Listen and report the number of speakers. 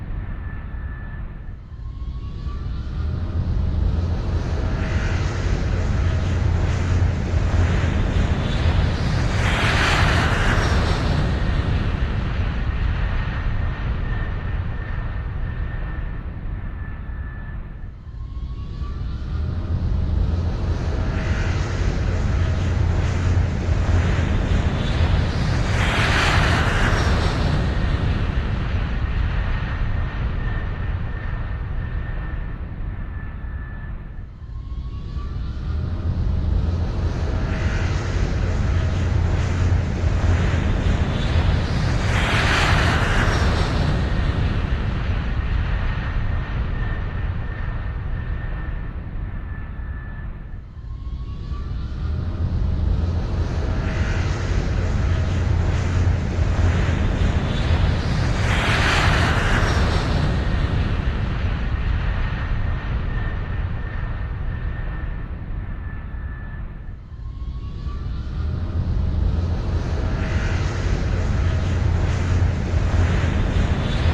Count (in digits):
0